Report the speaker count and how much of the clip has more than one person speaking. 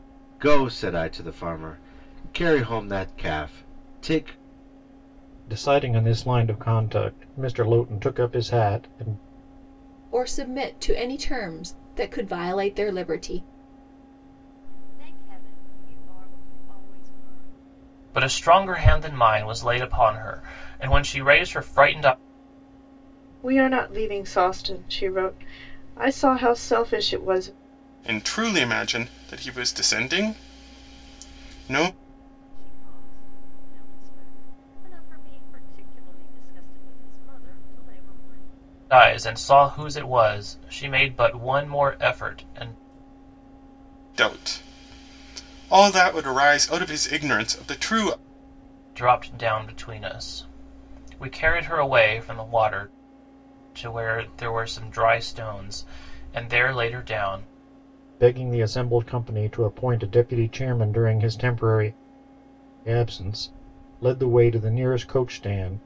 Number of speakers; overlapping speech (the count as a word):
seven, no overlap